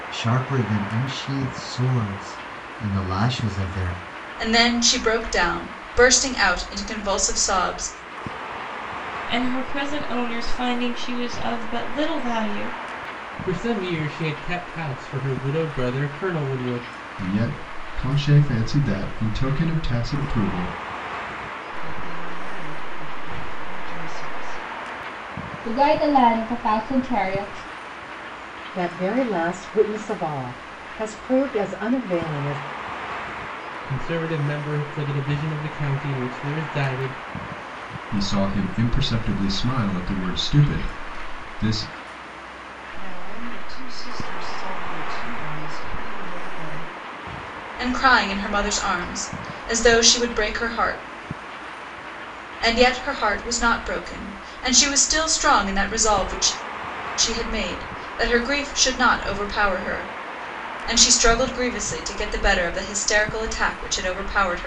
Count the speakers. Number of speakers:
8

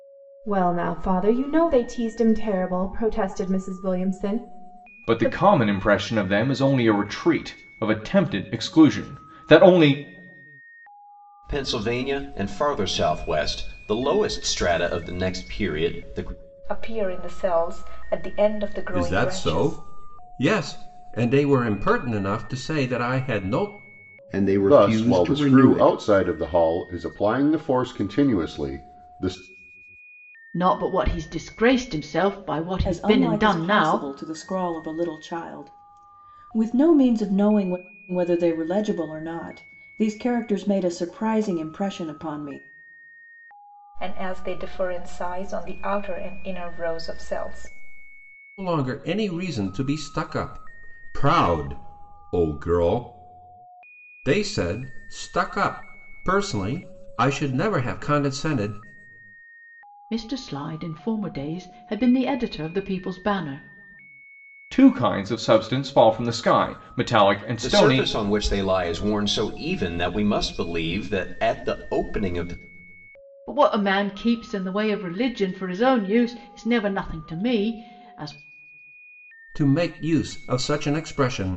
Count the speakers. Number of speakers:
9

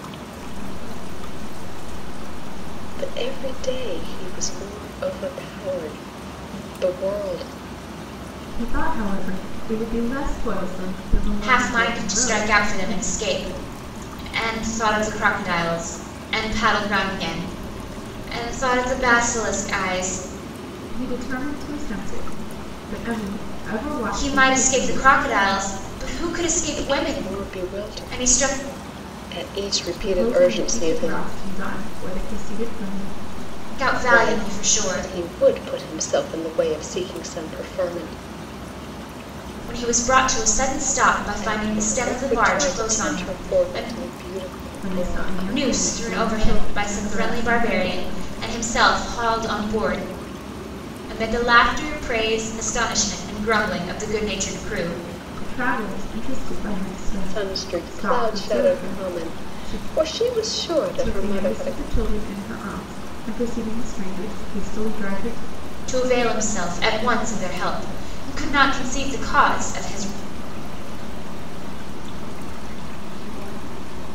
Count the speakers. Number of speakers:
4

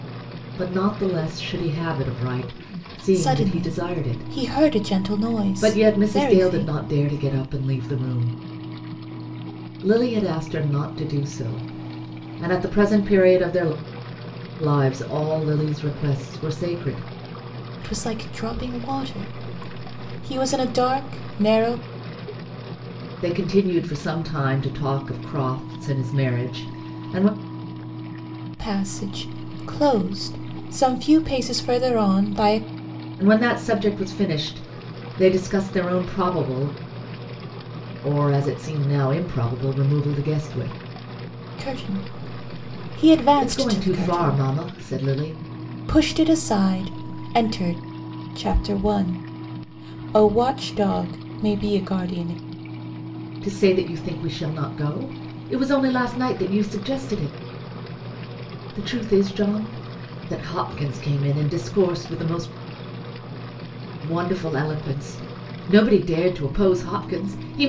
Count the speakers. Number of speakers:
2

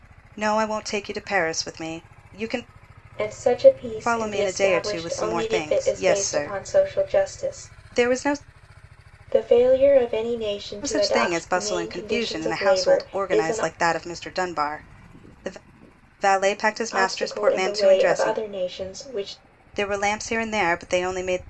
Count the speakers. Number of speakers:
2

